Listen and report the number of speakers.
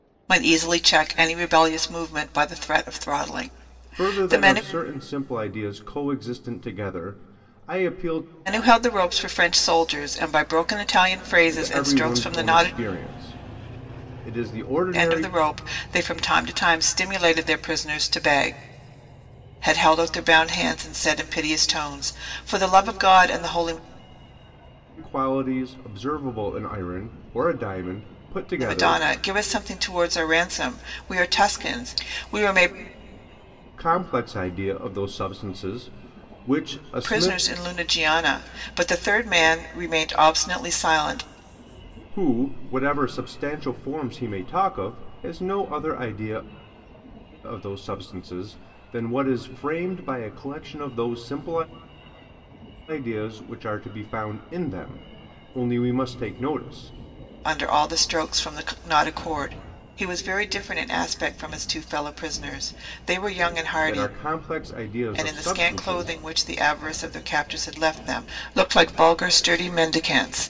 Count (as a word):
two